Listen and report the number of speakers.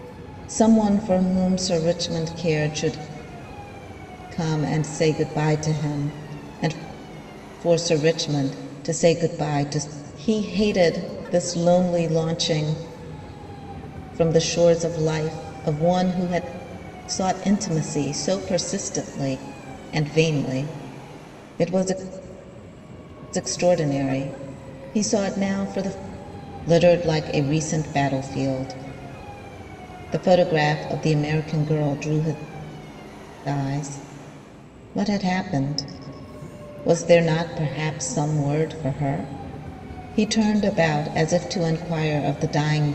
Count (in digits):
1